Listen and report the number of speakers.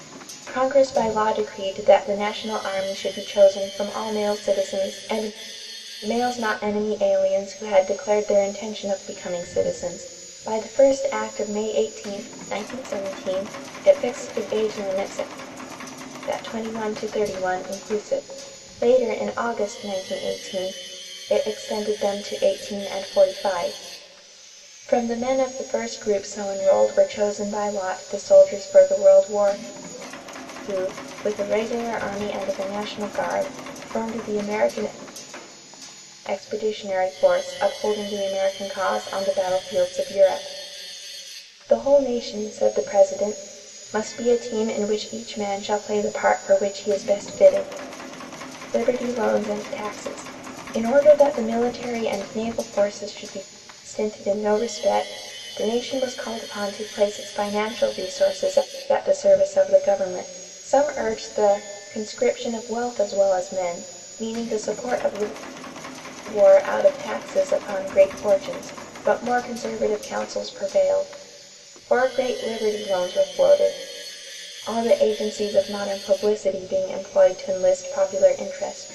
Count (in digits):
1